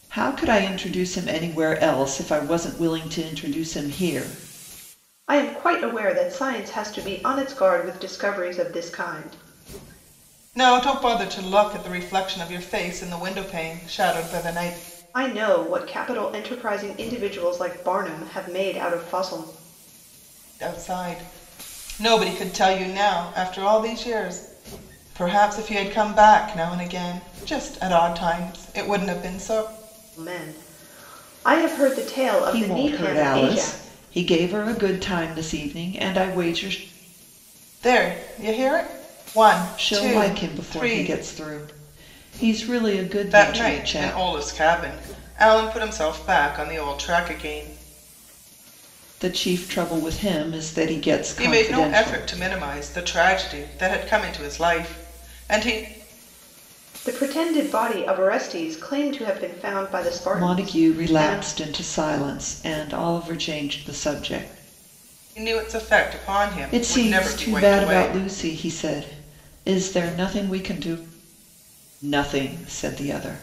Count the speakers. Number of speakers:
three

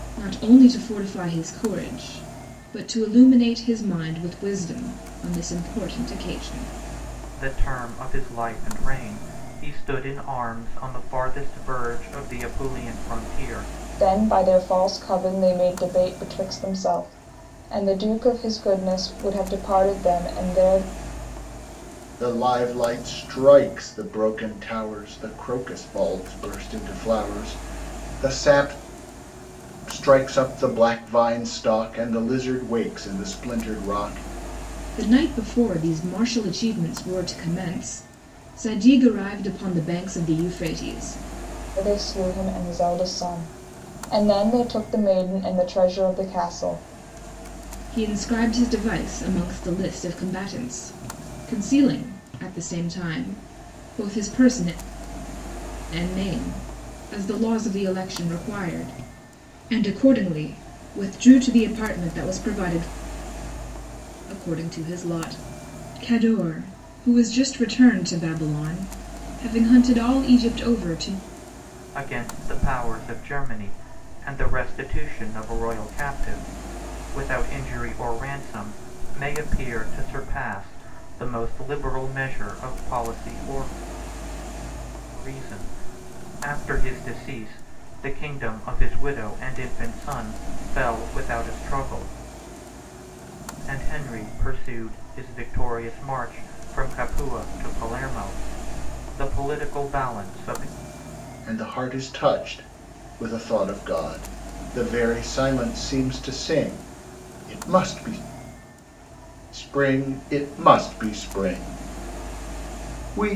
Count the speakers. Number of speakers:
four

